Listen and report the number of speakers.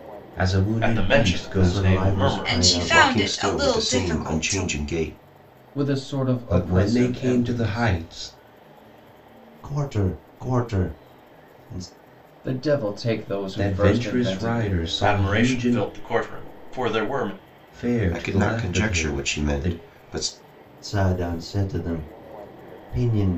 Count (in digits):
6